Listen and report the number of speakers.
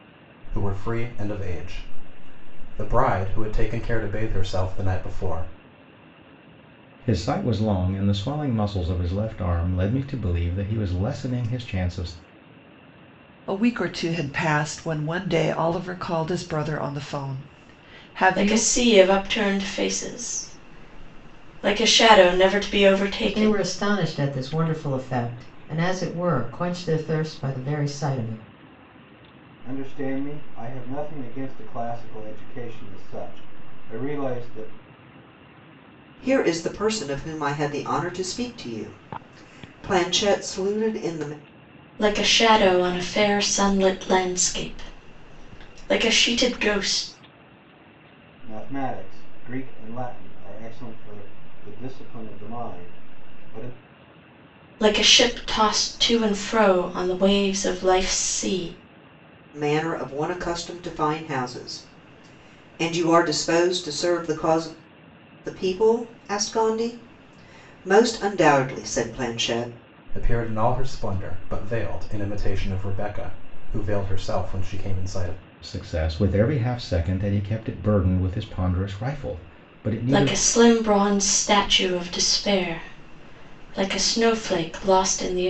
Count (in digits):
7